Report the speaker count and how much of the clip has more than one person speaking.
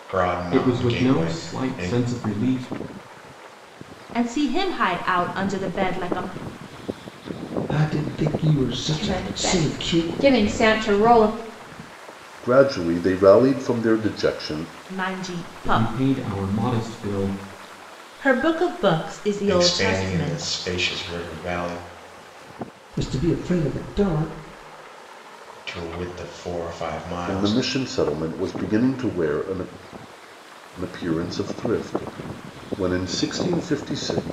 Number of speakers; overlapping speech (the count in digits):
6, about 13%